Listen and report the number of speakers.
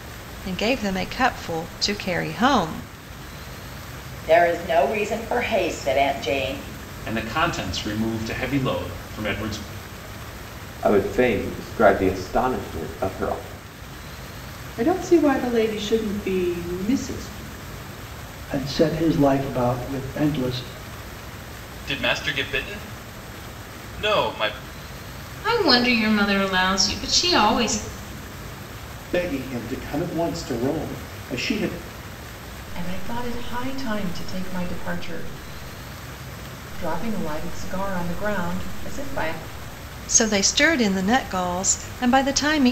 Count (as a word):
ten